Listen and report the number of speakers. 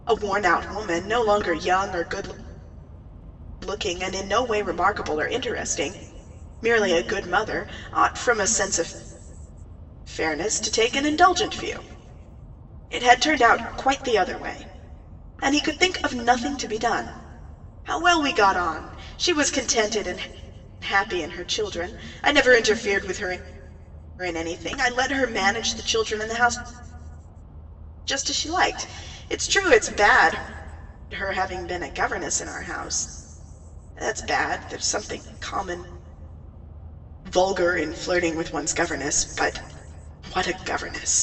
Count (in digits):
1